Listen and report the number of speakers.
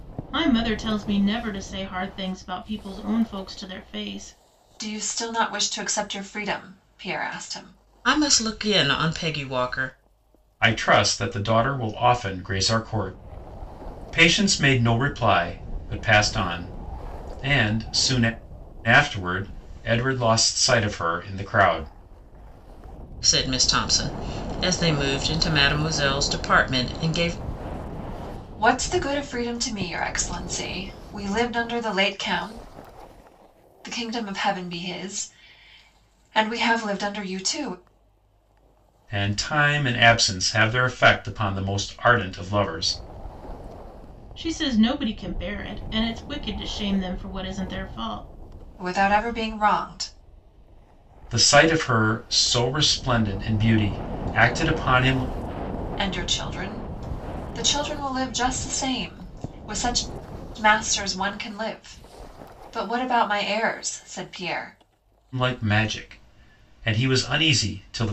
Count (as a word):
four